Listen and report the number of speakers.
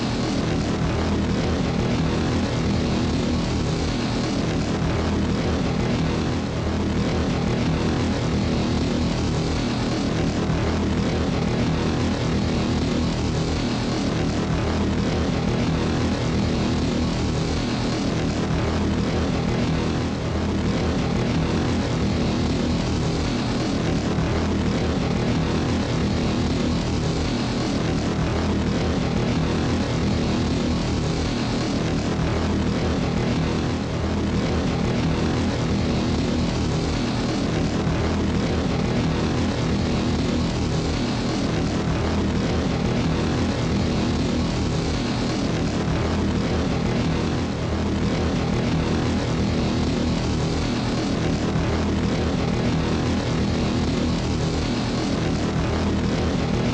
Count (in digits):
0